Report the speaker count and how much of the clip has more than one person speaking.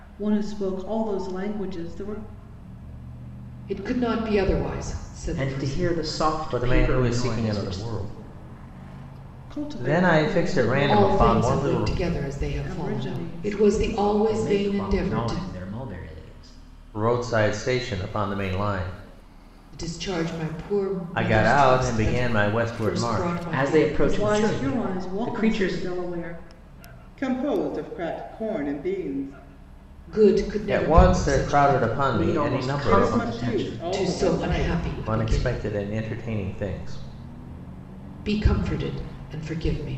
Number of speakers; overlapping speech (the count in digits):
4, about 39%